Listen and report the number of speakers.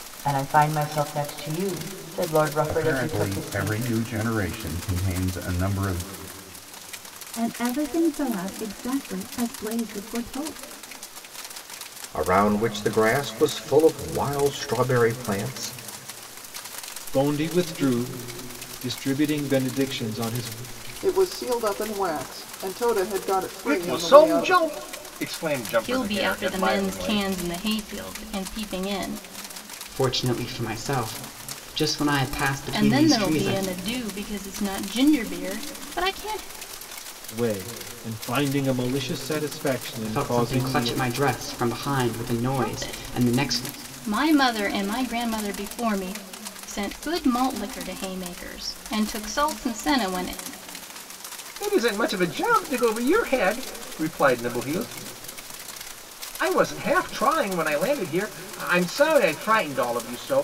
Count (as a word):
nine